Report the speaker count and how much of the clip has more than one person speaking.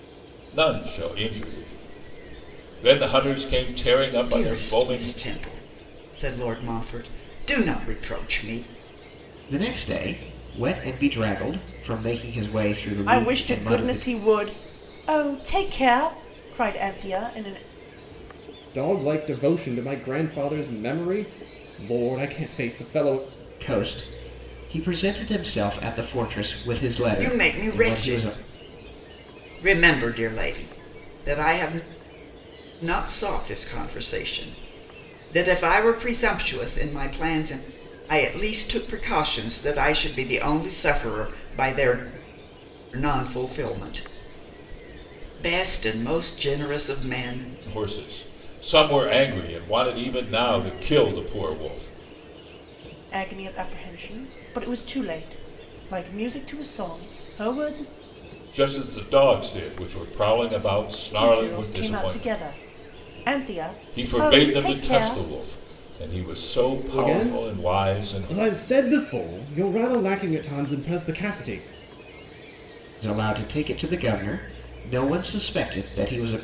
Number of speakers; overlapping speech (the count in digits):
5, about 9%